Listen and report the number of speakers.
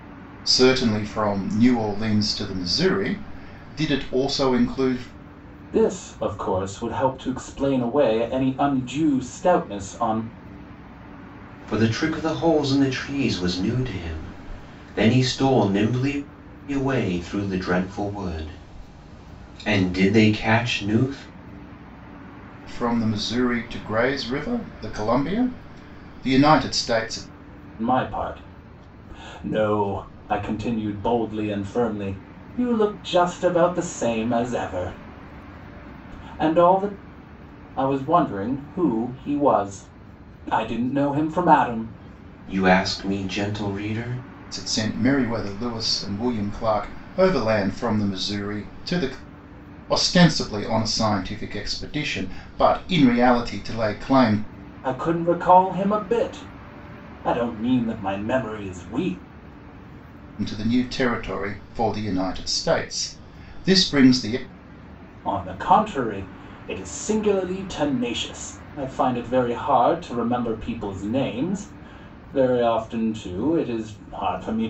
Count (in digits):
3